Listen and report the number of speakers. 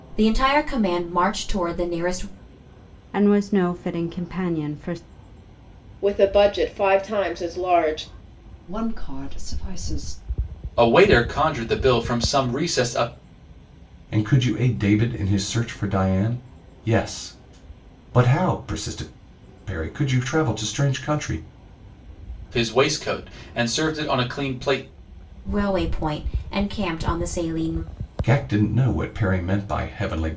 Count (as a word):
six